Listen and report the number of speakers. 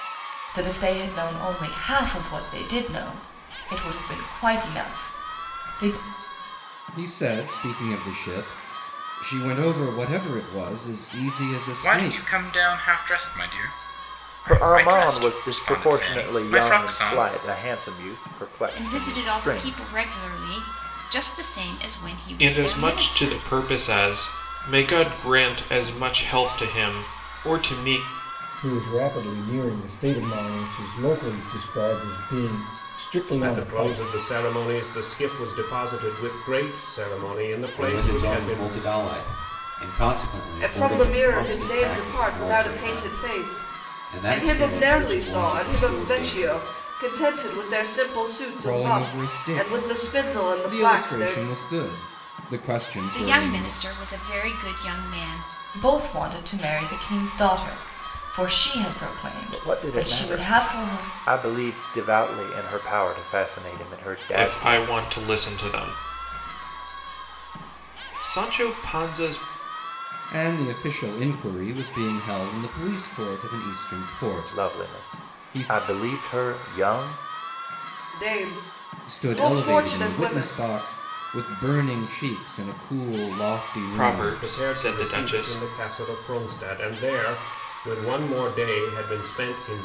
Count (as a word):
ten